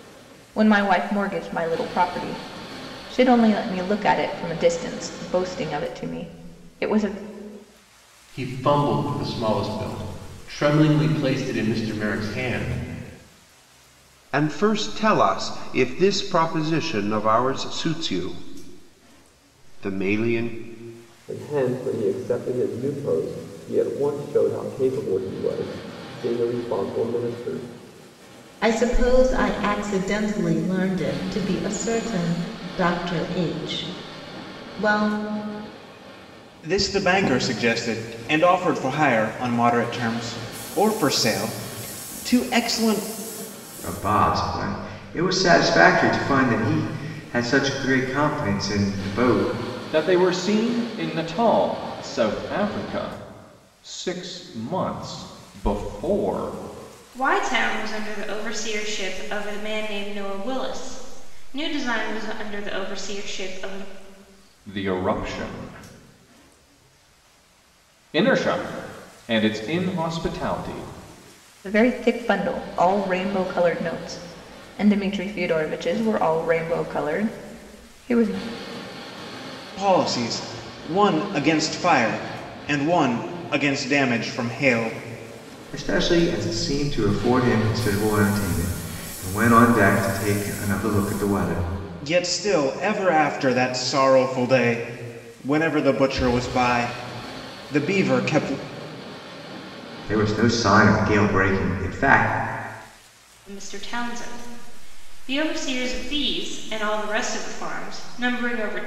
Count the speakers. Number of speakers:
9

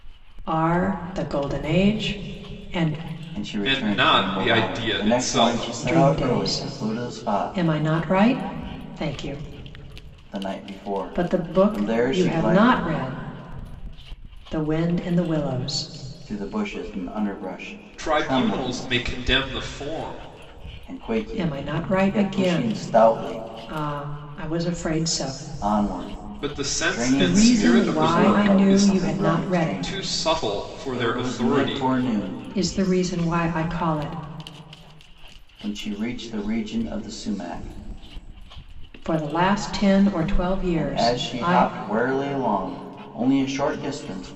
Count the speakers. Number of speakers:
3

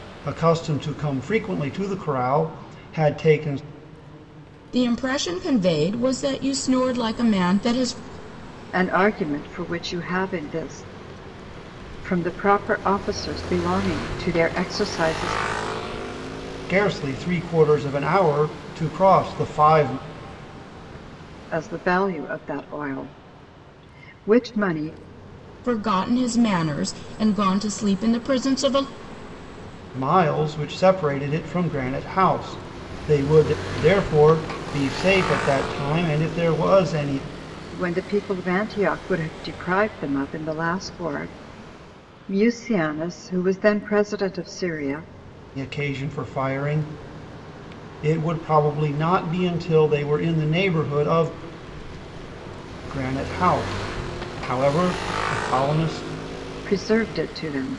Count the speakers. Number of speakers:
3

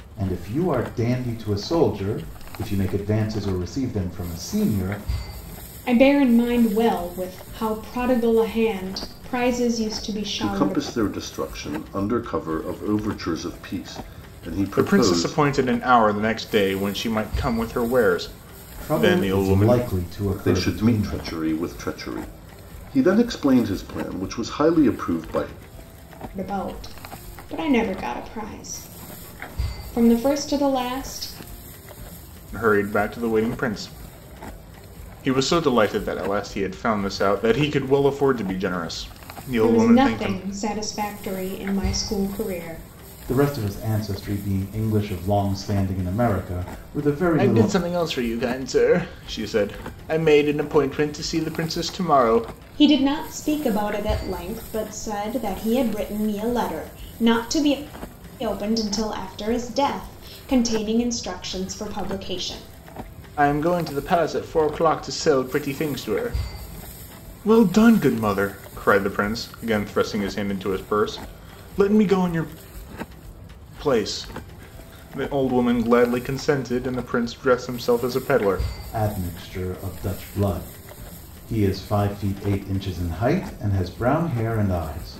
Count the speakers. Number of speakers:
4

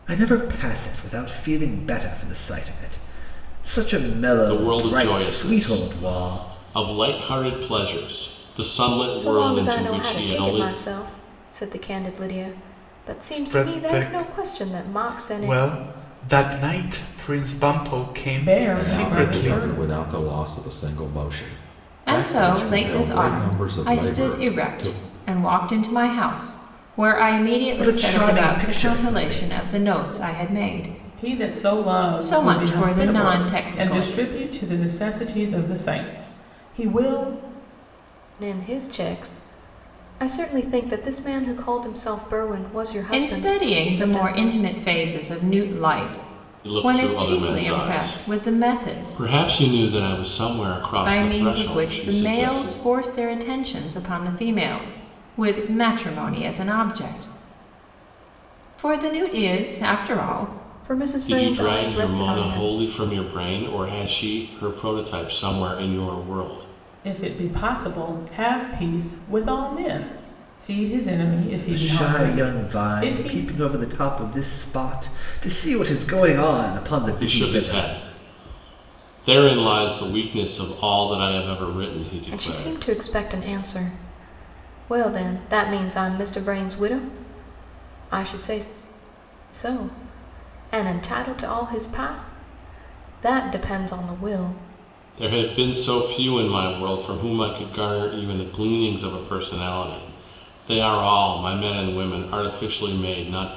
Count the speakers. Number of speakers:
7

